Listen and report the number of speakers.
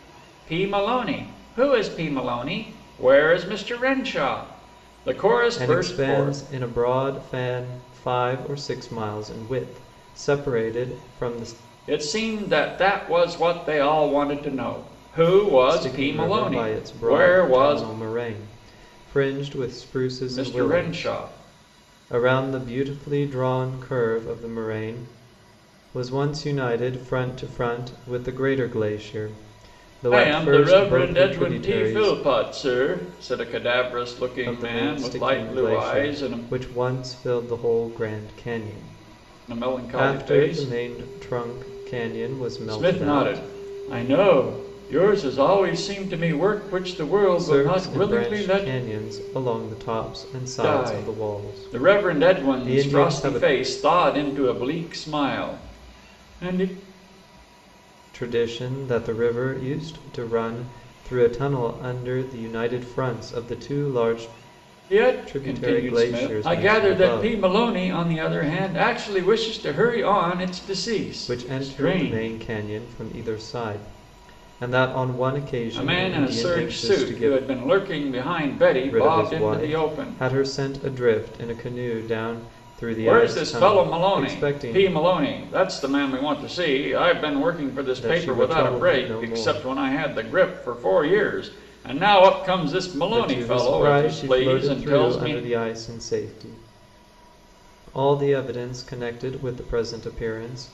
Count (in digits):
2